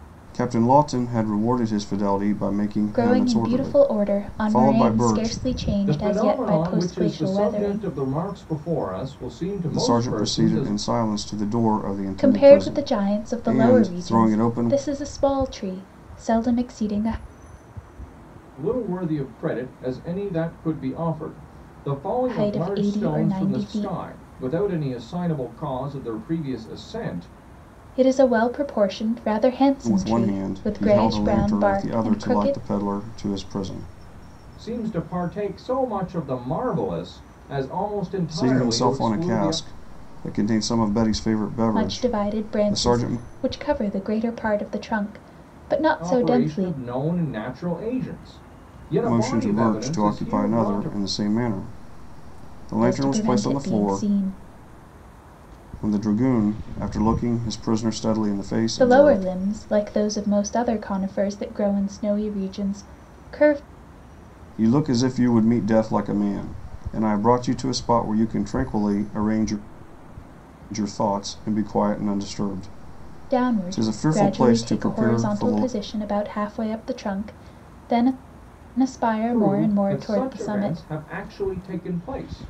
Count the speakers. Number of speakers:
3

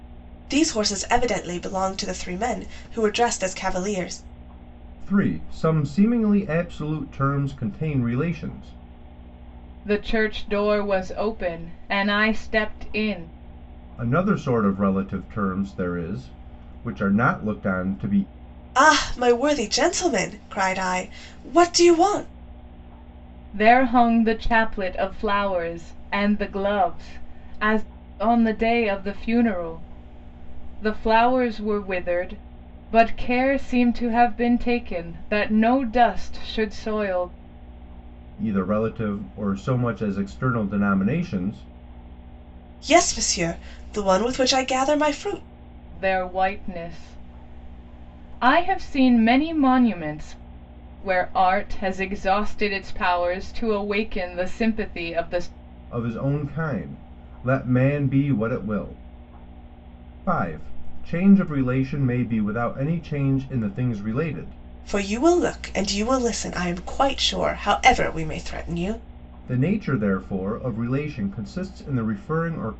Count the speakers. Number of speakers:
3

